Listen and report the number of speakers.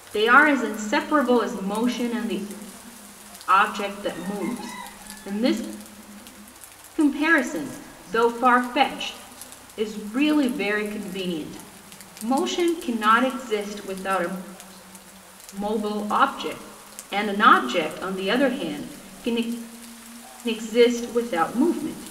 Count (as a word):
one